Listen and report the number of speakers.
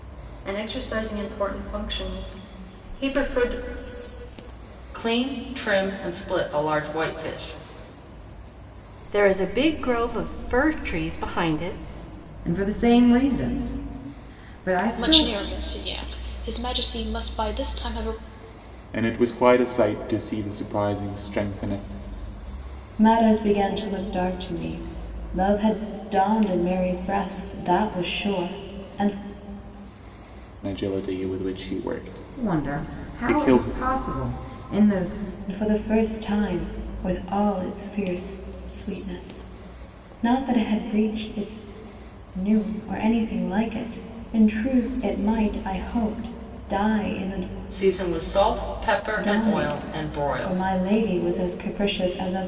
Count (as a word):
seven